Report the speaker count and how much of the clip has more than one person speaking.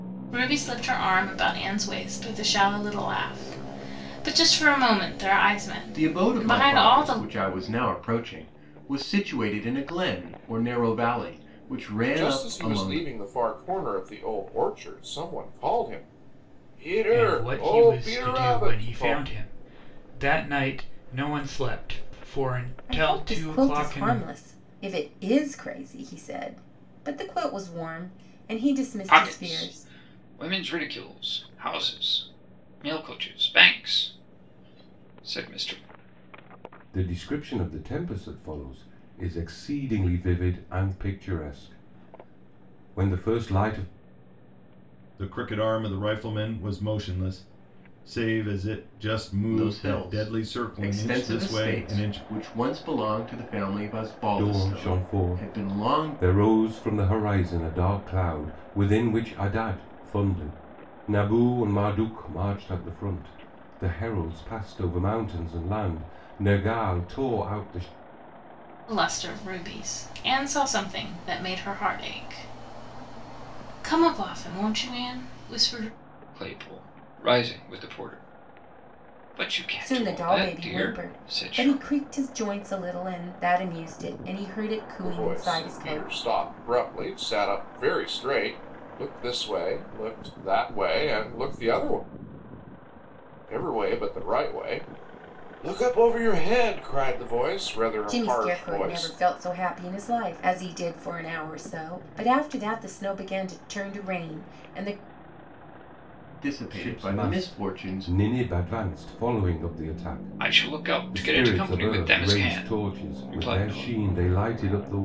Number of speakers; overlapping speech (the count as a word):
eight, about 18%